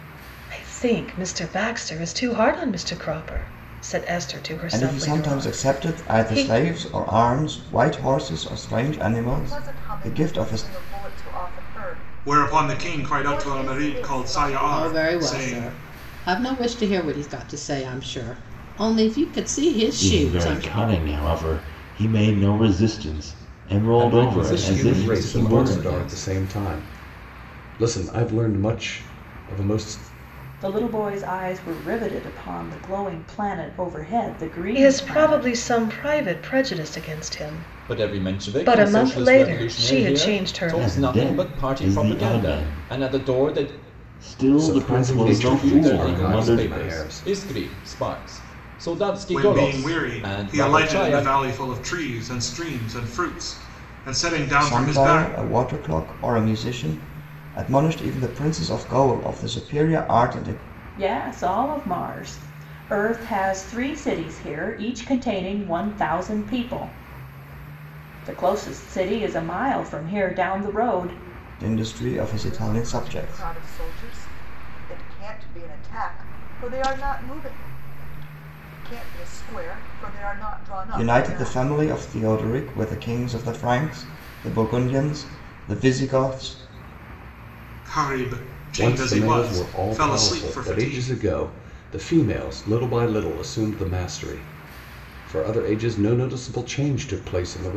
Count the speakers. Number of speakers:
9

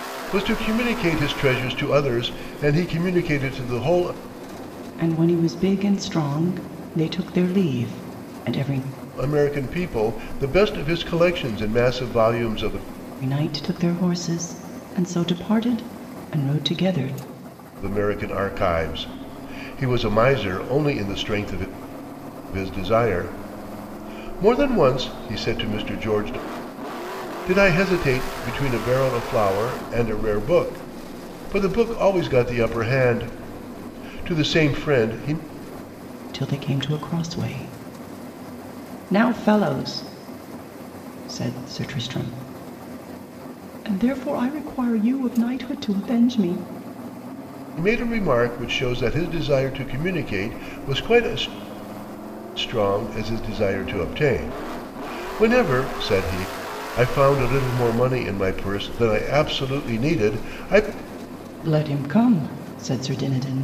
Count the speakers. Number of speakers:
2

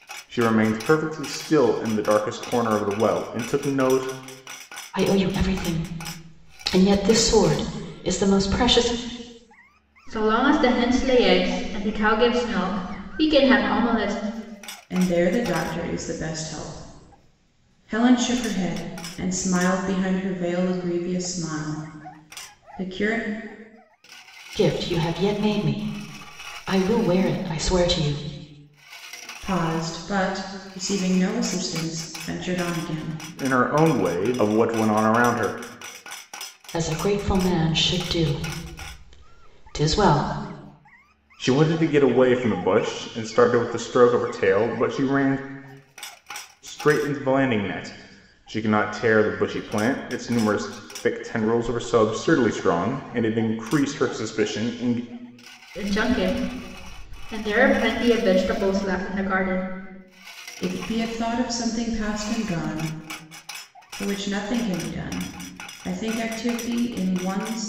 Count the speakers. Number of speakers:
4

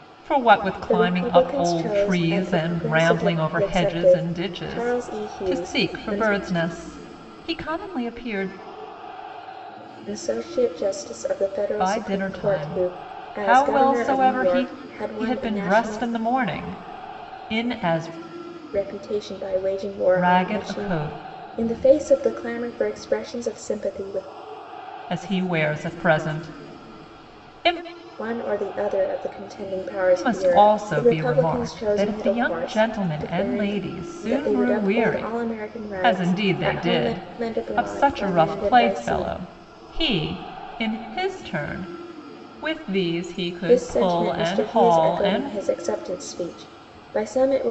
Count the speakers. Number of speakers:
2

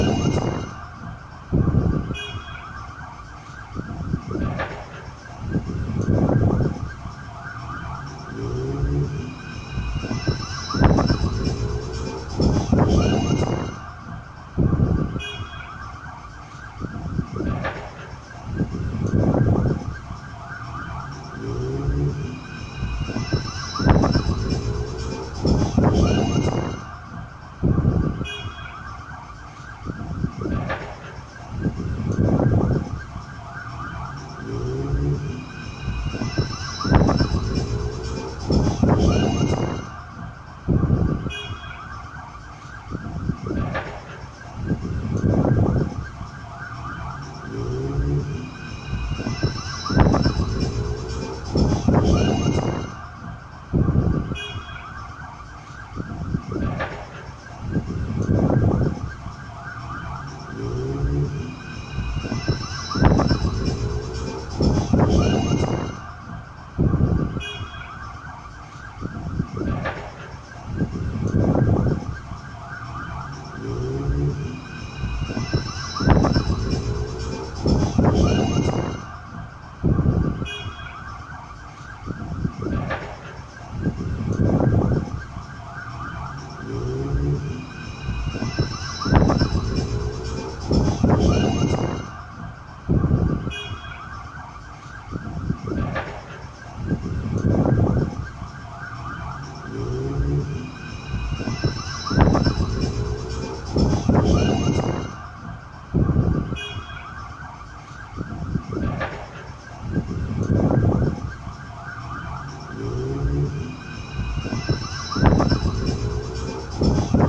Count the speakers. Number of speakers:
0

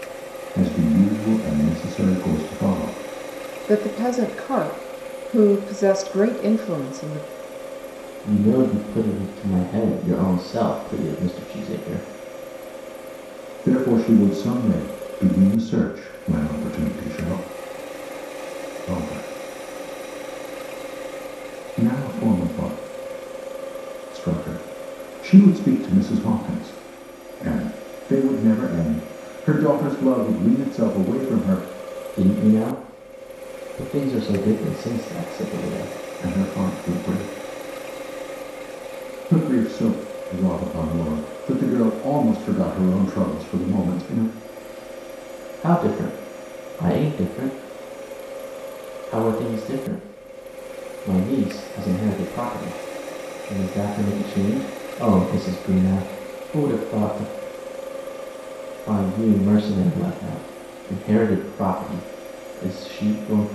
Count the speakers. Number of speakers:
3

